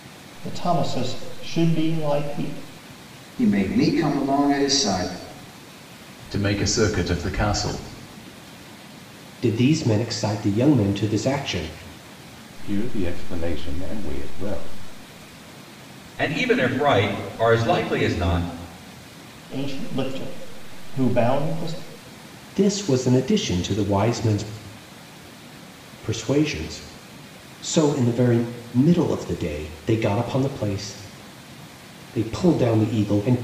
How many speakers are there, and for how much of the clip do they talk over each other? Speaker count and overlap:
6, no overlap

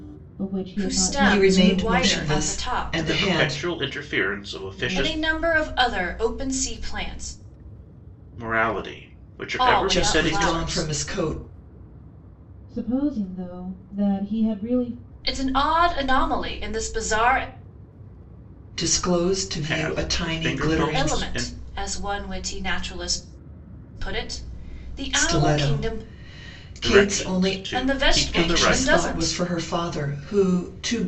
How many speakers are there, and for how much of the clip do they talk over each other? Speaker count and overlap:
4, about 32%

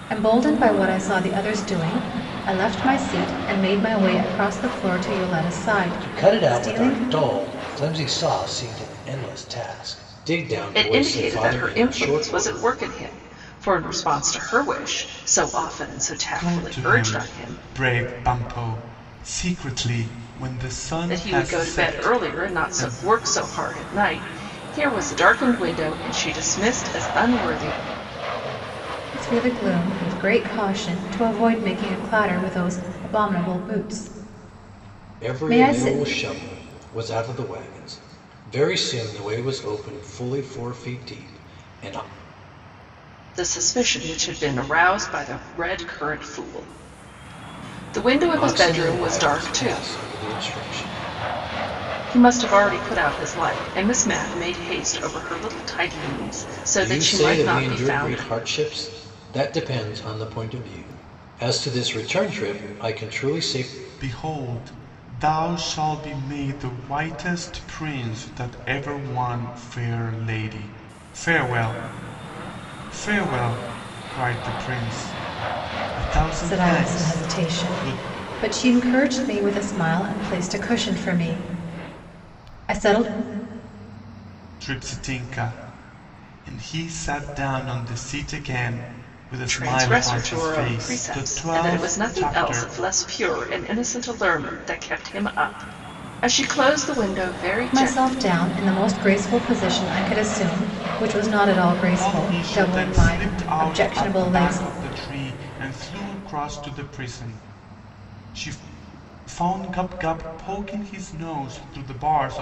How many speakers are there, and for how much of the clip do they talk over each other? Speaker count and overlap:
4, about 17%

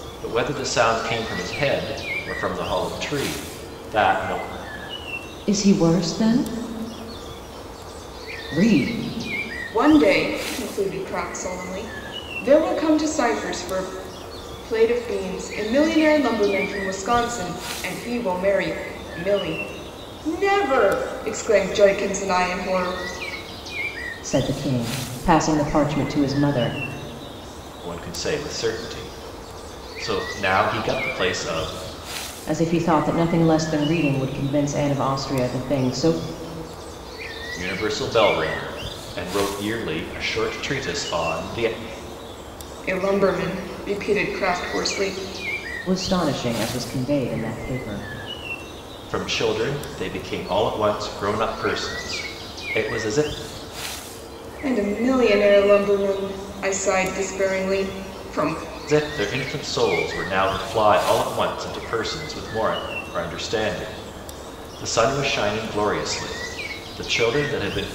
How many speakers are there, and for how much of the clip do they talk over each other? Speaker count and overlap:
3, no overlap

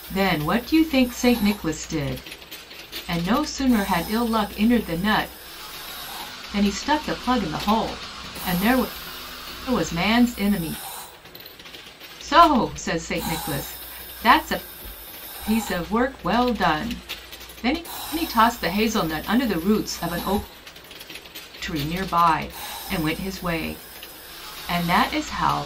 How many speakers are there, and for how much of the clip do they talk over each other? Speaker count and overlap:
1, no overlap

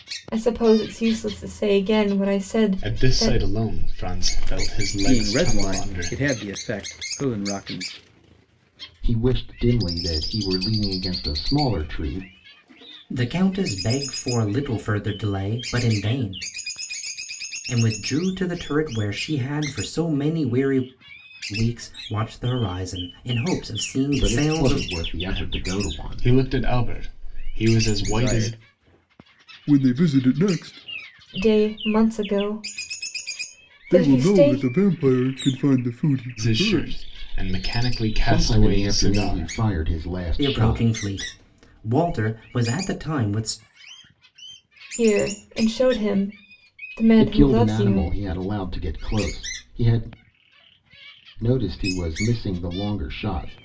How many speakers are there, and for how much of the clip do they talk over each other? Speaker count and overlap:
5, about 16%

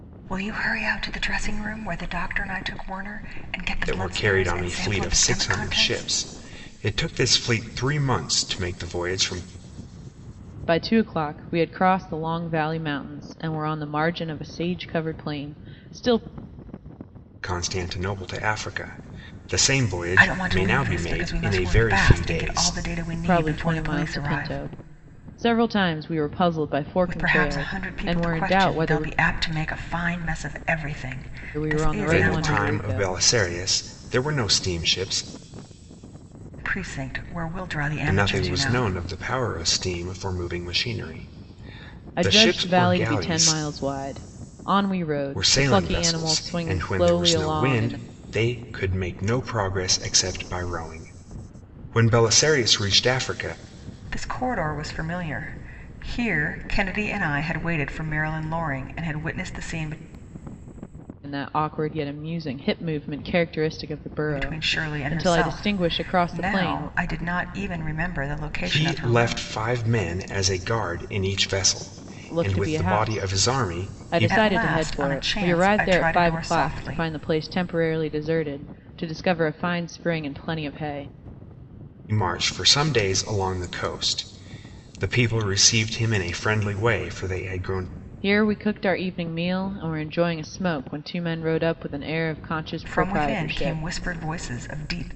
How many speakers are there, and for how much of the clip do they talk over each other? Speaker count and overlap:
3, about 26%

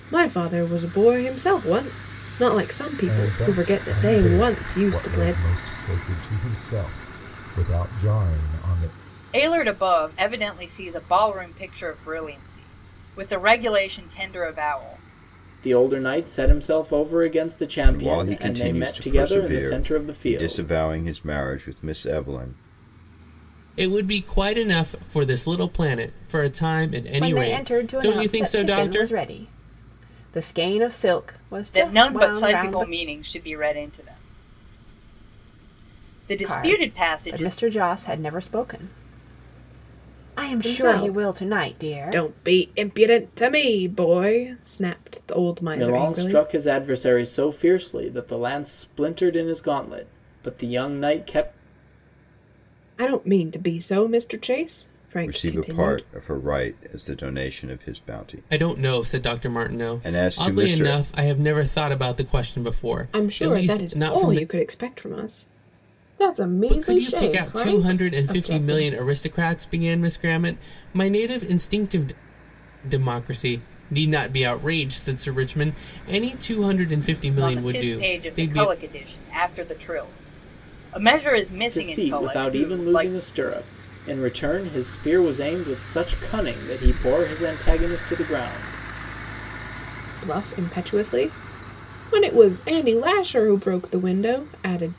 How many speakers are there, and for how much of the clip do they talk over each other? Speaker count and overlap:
7, about 23%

